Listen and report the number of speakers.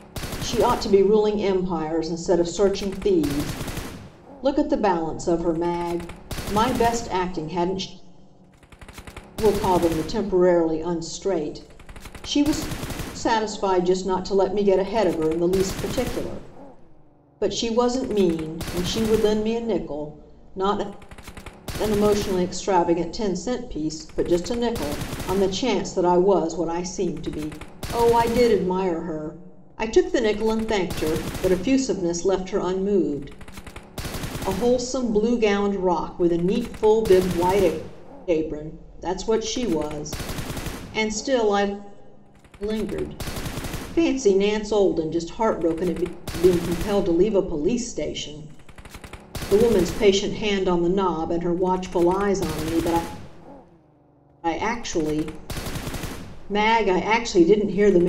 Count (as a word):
one